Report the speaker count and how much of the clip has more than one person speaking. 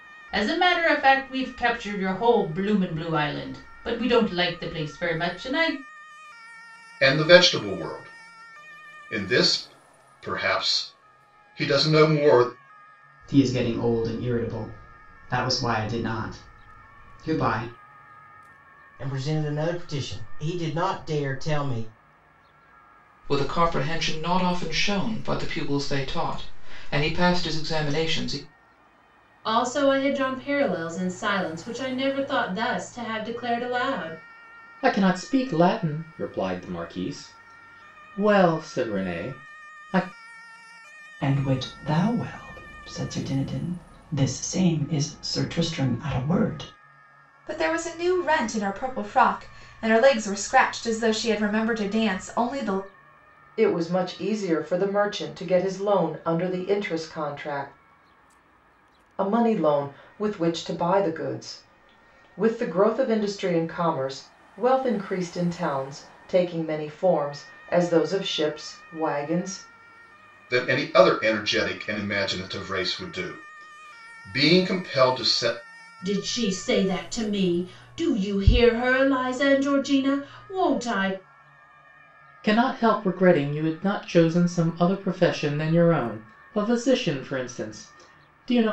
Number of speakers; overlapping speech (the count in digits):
10, no overlap